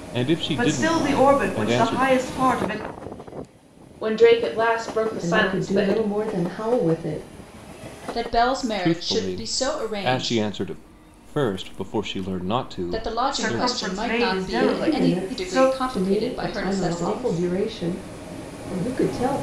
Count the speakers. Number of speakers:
5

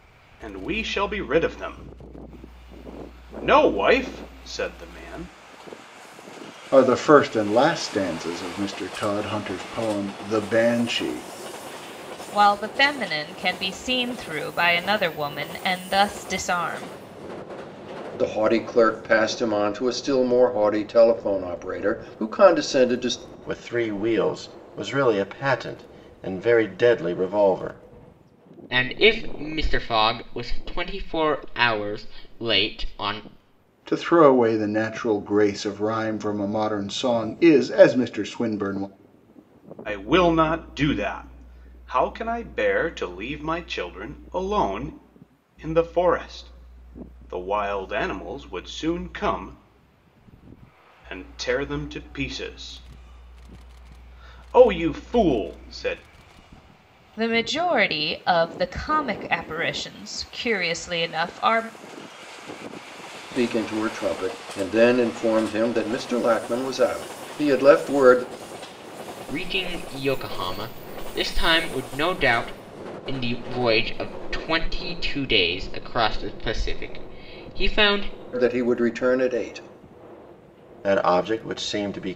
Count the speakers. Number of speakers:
6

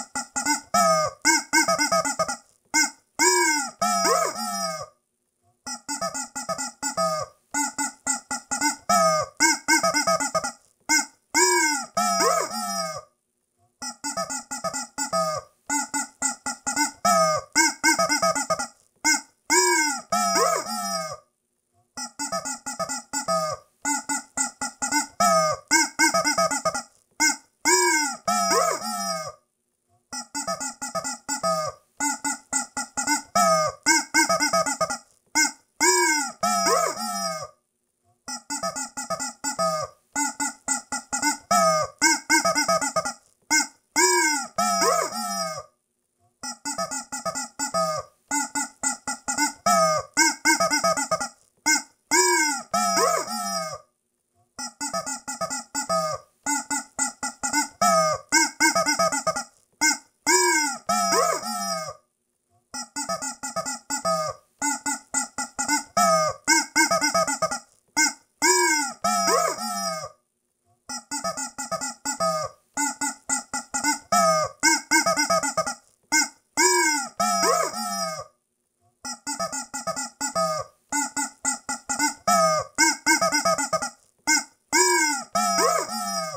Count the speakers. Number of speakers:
0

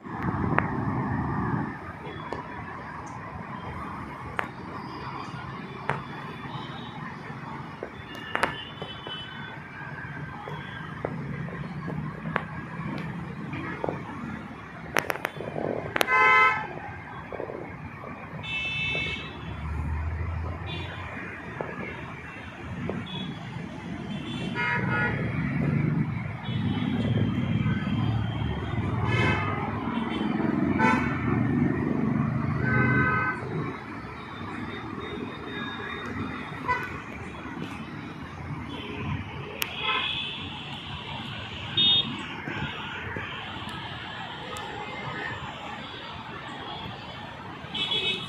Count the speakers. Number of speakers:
0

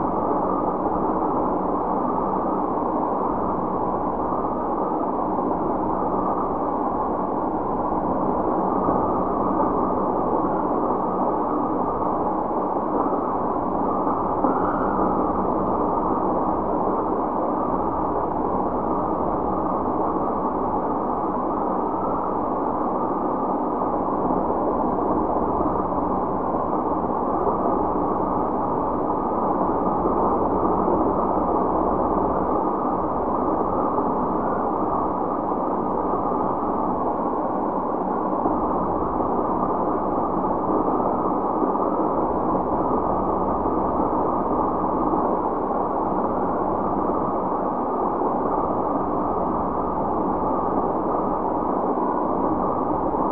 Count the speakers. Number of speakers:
0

